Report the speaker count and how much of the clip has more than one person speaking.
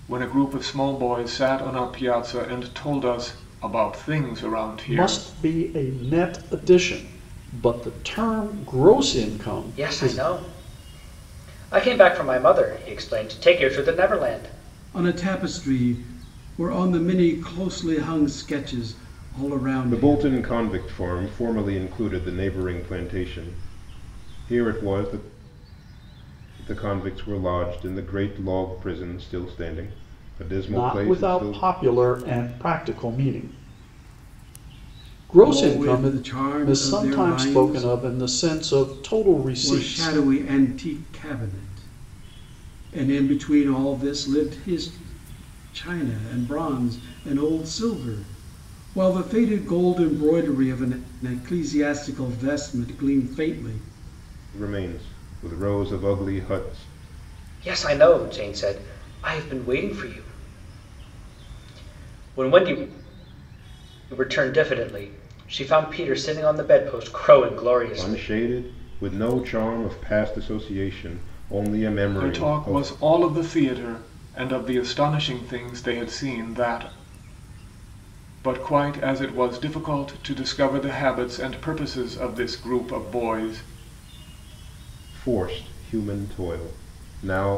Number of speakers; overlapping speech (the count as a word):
five, about 7%